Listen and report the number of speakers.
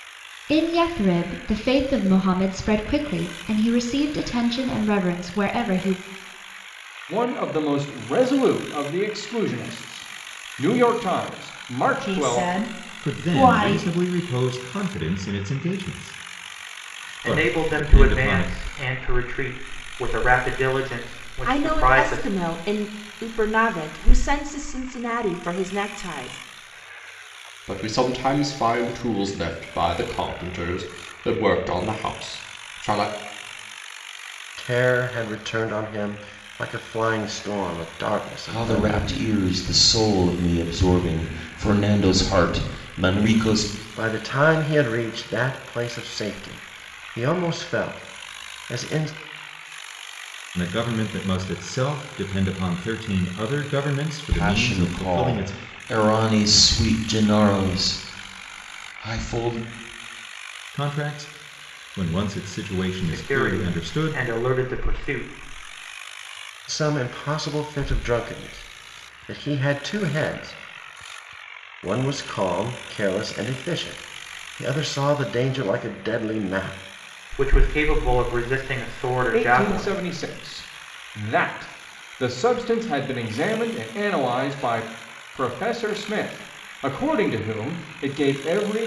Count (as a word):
nine